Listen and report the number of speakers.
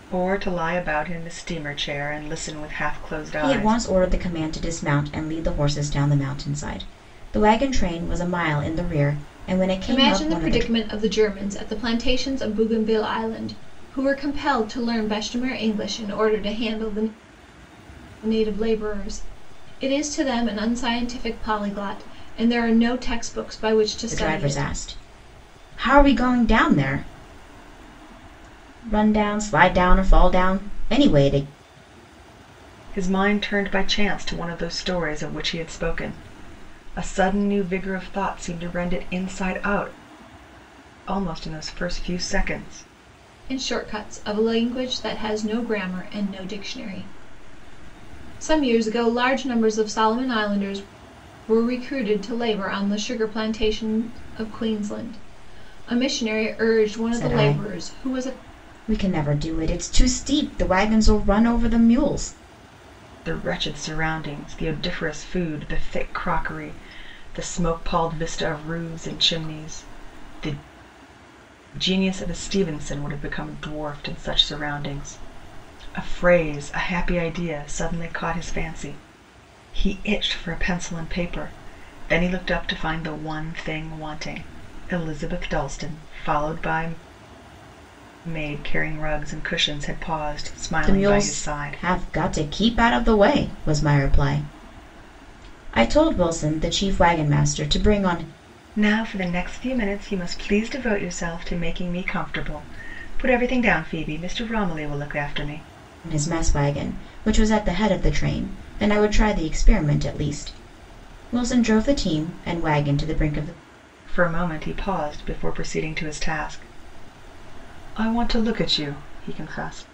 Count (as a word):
three